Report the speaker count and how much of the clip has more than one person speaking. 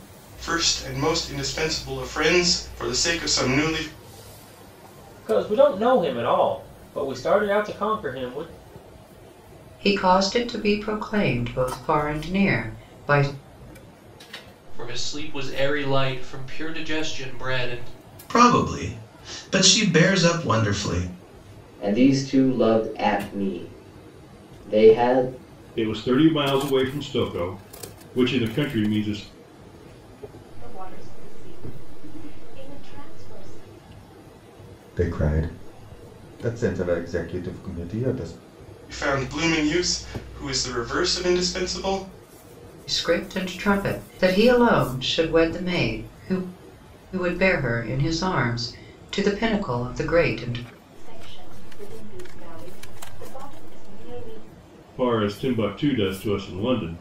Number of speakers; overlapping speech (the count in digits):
9, no overlap